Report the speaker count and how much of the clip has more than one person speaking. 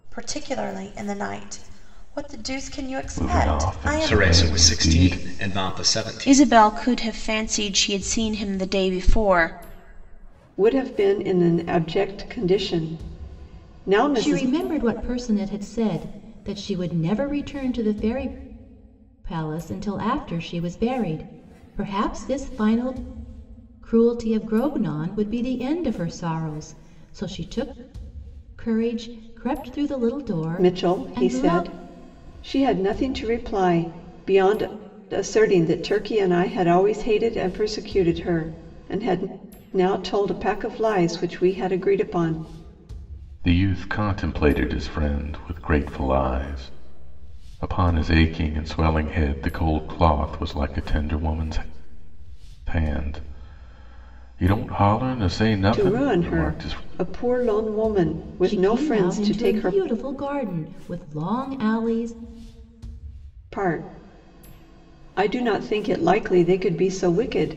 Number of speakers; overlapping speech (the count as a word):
six, about 10%